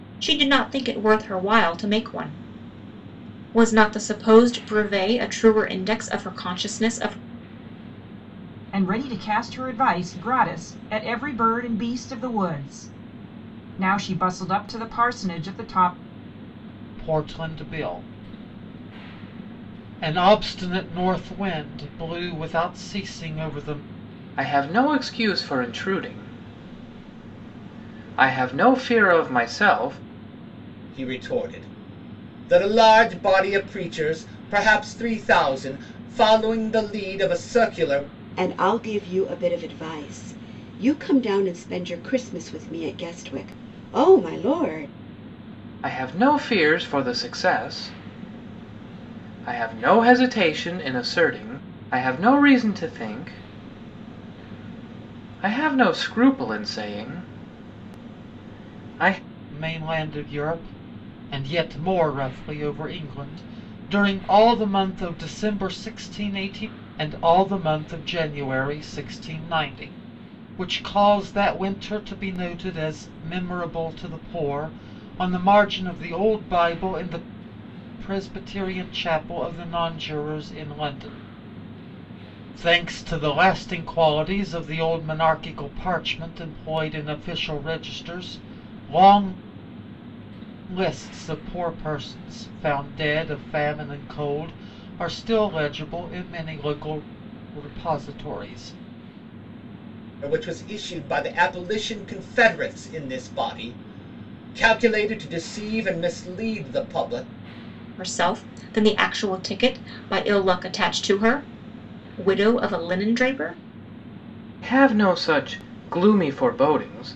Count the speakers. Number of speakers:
six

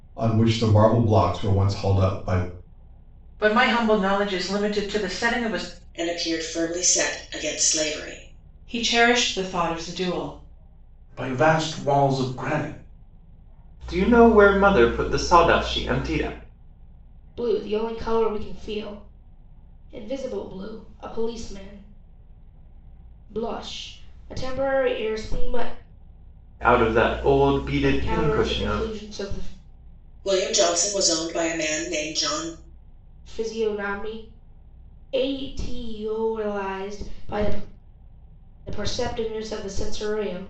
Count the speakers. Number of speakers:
seven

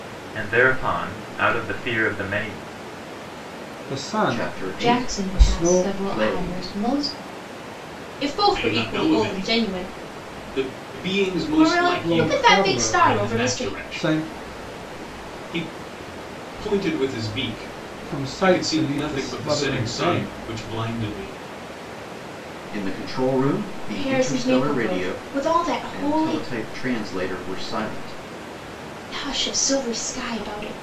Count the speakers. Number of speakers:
six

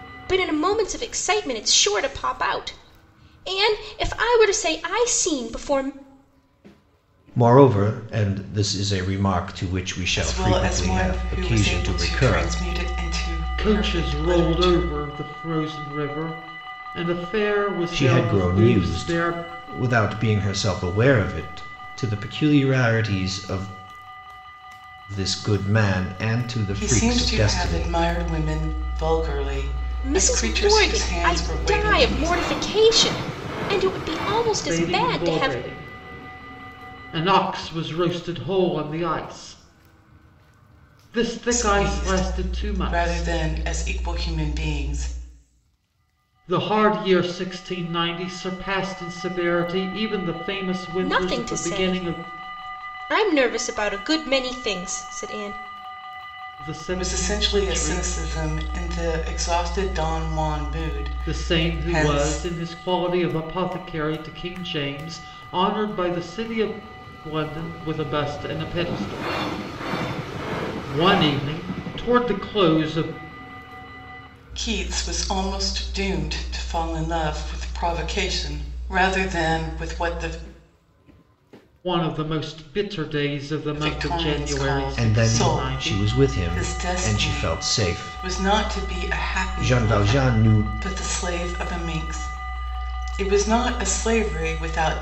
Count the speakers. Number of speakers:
four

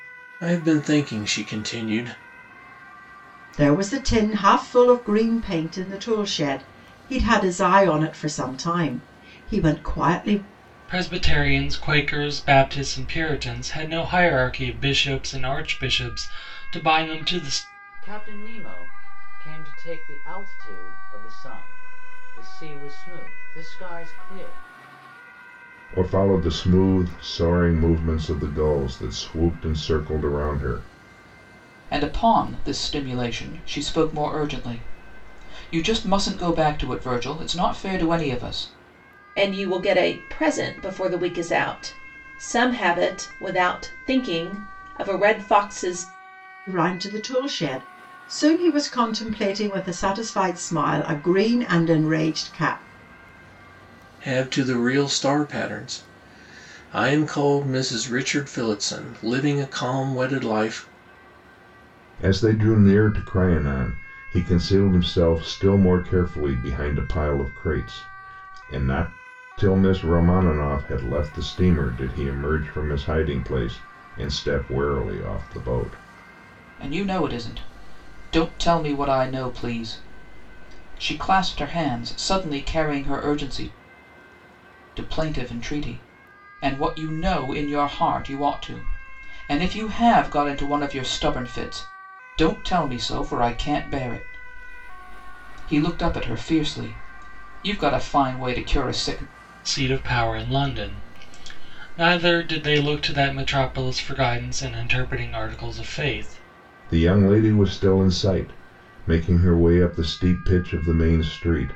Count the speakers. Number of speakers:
seven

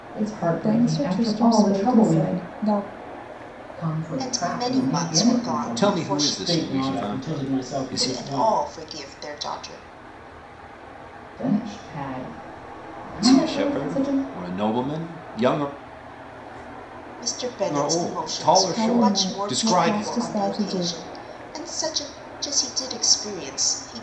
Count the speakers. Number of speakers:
six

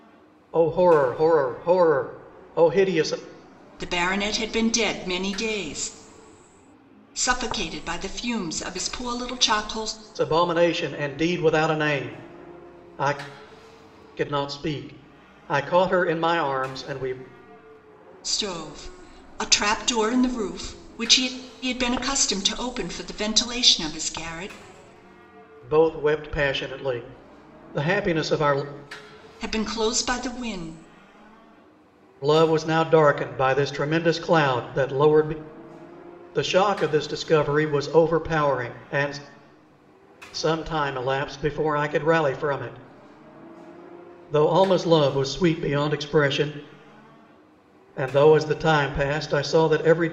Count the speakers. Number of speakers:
two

